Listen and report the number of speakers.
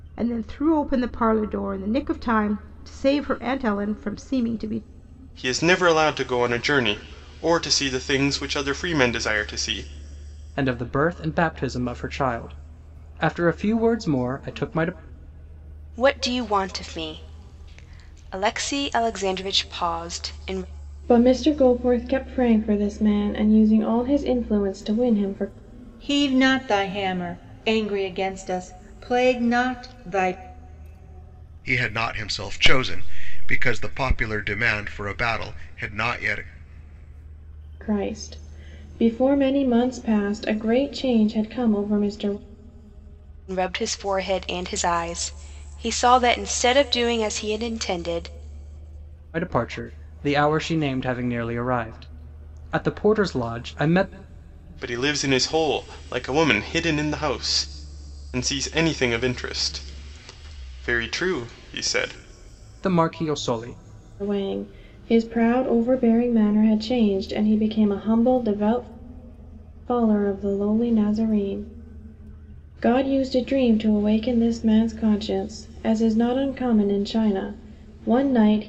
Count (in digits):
7